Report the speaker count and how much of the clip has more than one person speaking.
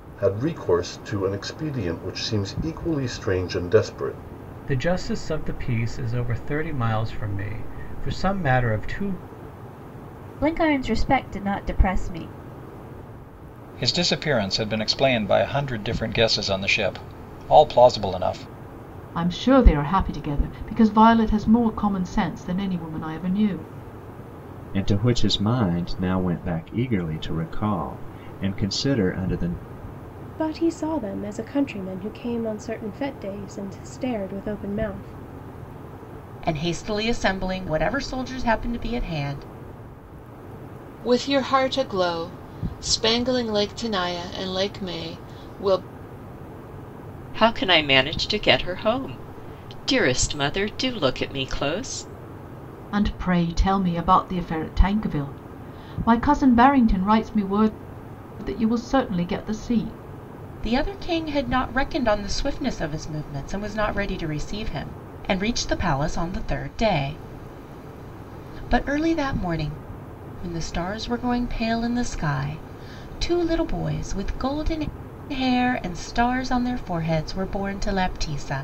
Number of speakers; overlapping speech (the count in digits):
10, no overlap